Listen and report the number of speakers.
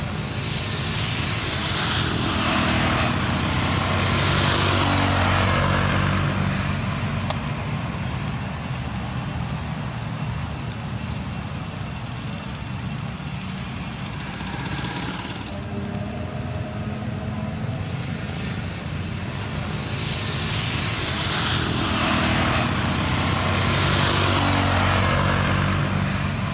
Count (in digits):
0